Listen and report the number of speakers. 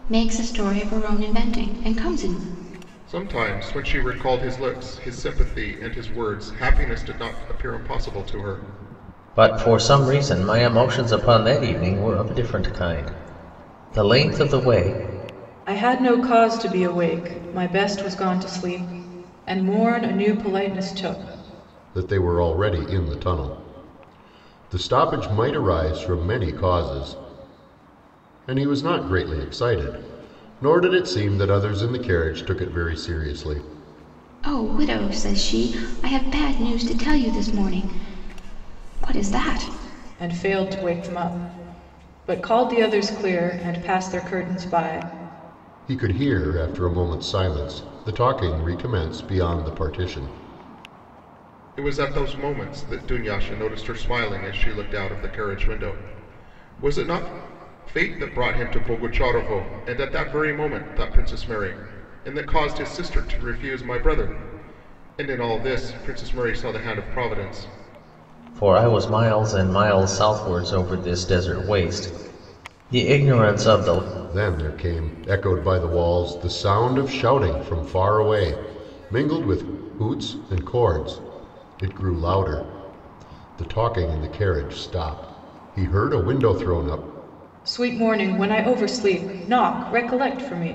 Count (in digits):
5